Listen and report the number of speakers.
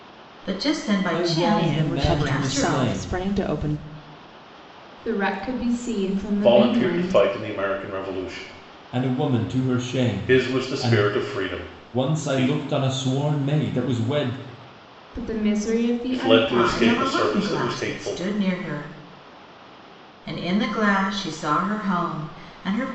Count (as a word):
five